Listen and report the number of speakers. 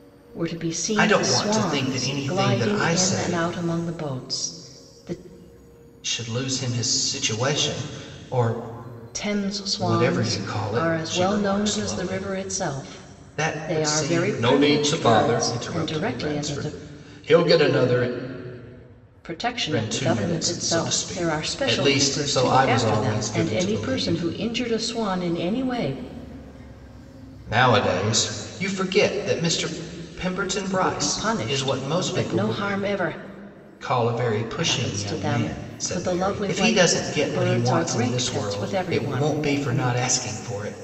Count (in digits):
2